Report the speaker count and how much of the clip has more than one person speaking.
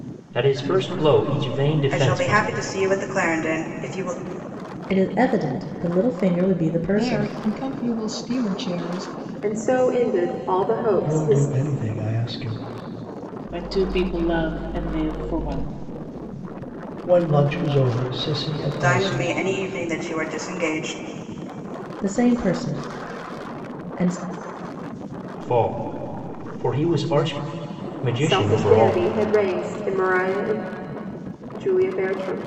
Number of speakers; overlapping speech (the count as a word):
seven, about 9%